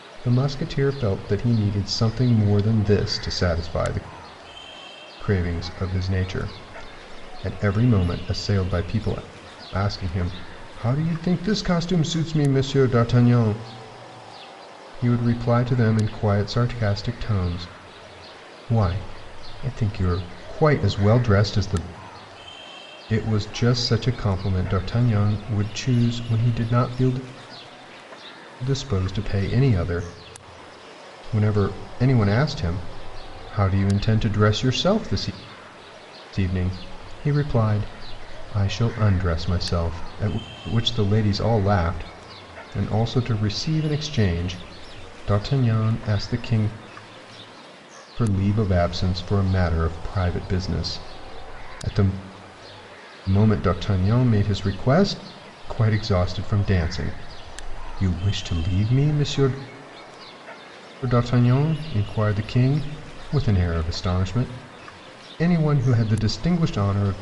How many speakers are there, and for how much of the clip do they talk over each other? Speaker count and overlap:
1, no overlap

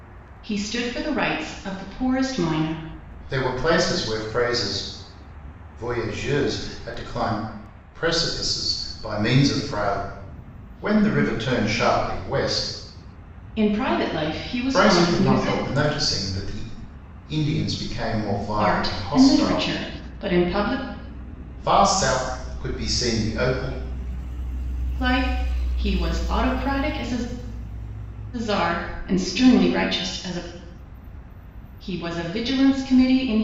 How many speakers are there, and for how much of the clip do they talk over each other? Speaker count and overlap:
2, about 7%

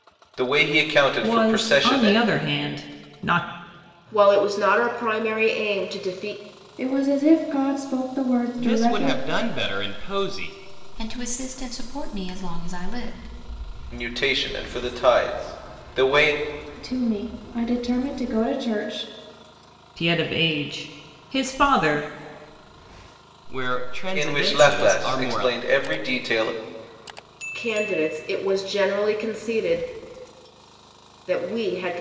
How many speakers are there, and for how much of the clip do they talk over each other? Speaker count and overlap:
6, about 10%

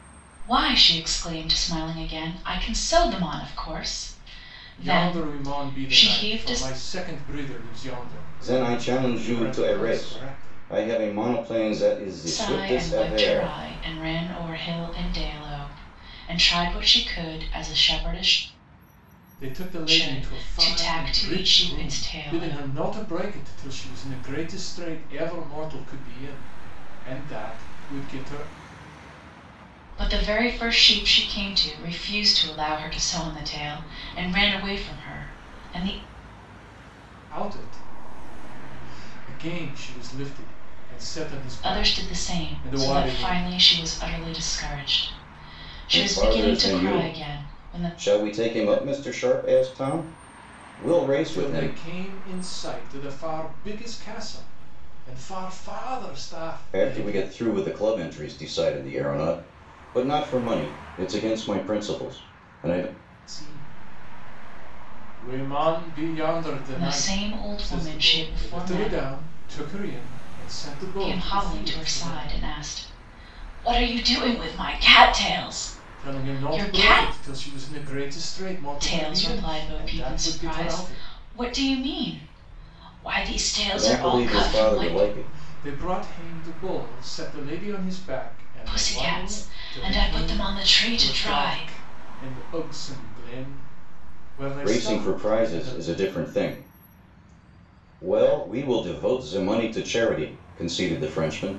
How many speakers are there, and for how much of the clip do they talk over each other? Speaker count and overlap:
3, about 26%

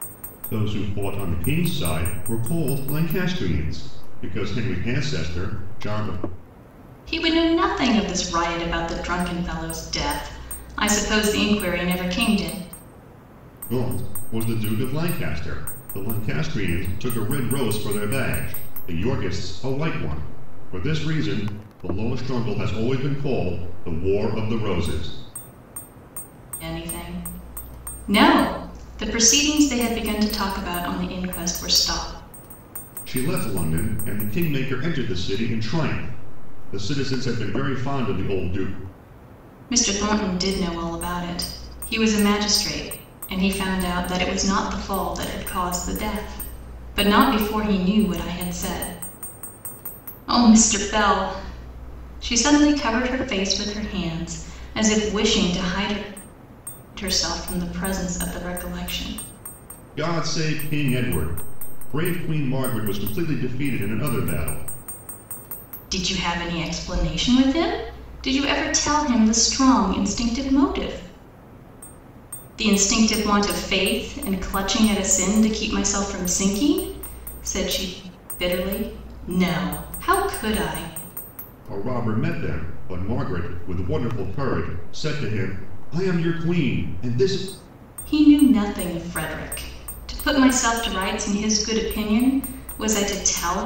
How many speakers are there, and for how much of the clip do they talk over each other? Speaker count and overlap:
2, no overlap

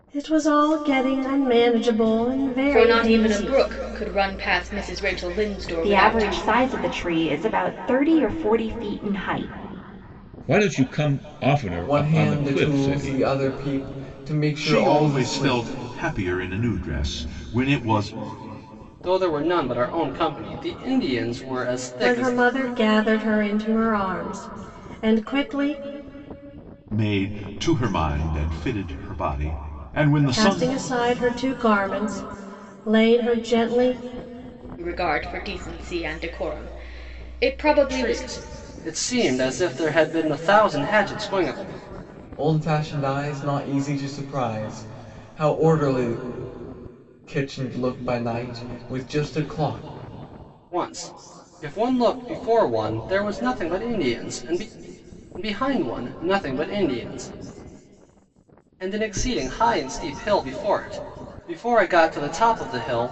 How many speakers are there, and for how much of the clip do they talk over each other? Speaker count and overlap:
7, about 9%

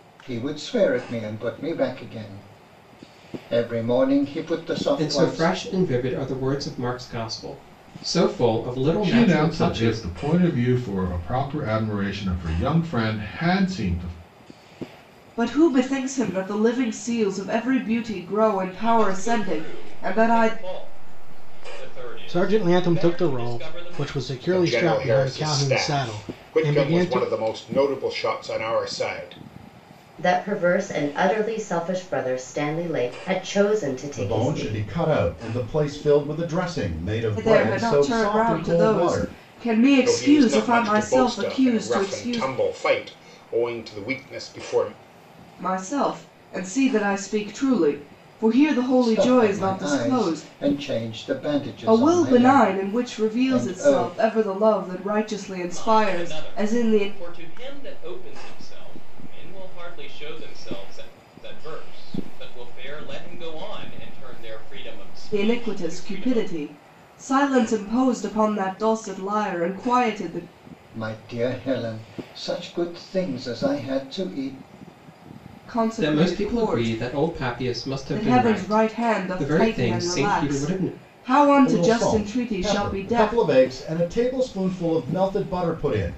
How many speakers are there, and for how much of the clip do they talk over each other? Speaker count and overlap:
9, about 30%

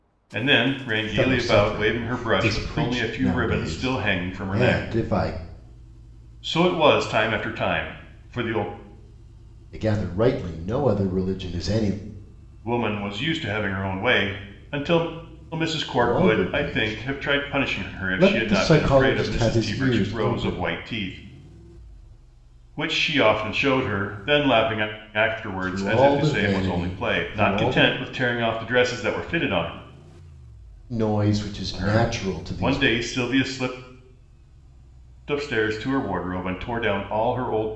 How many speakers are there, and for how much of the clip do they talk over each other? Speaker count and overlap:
2, about 32%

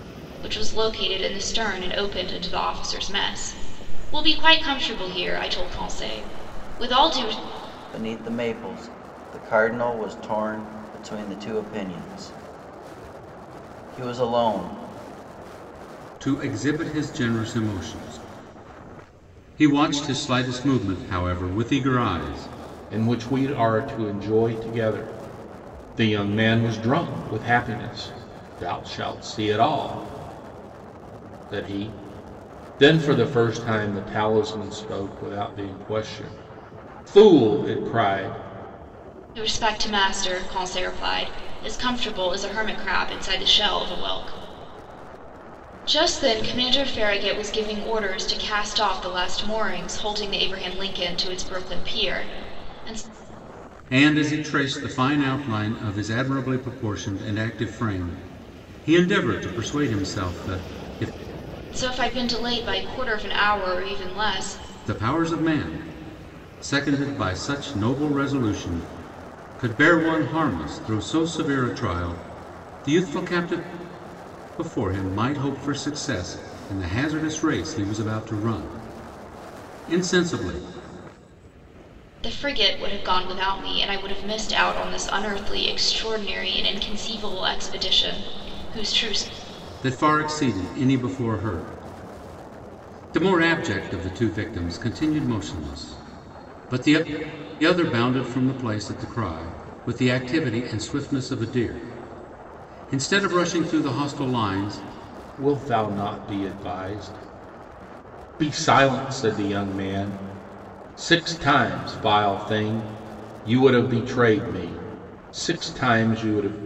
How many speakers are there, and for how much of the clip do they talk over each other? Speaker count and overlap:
4, no overlap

